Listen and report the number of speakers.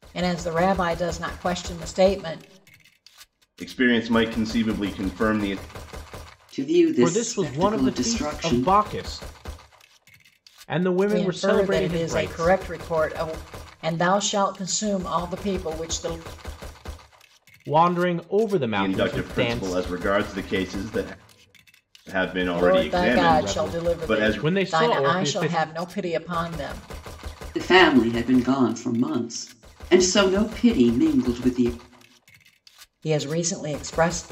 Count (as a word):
four